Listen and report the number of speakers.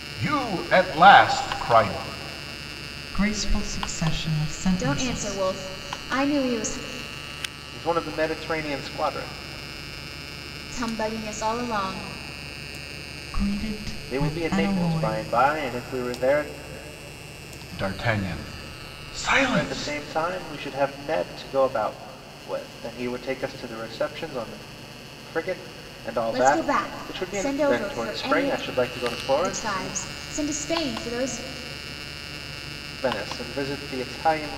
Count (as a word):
four